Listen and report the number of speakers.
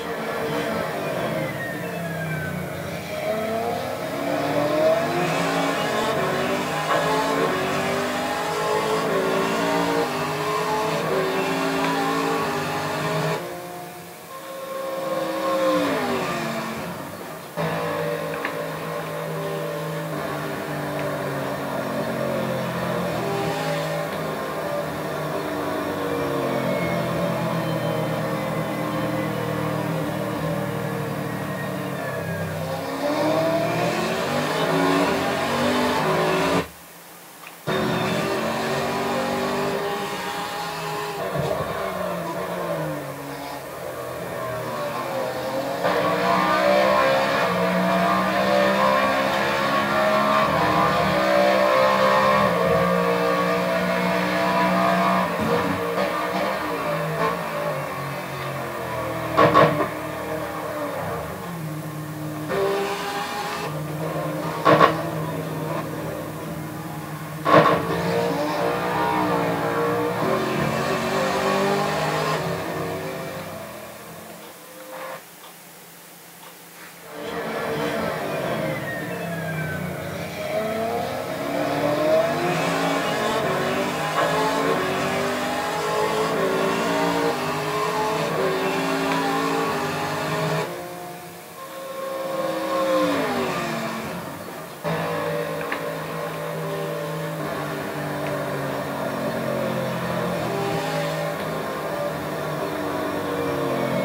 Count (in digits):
0